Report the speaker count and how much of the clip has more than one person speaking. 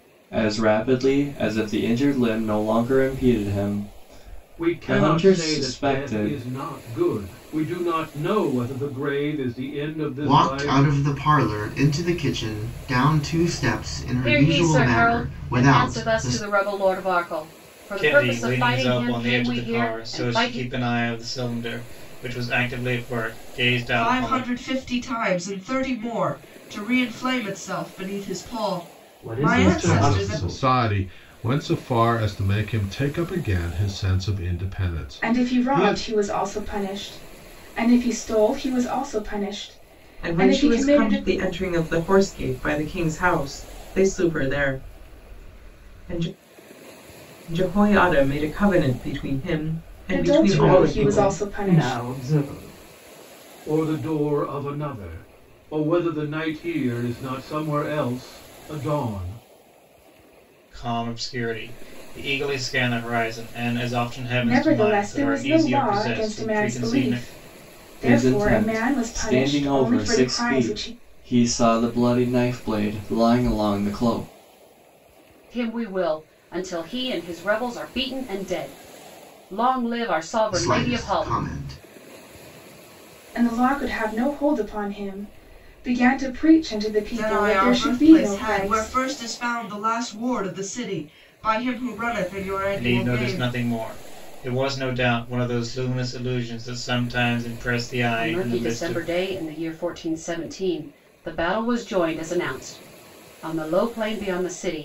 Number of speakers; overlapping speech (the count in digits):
10, about 23%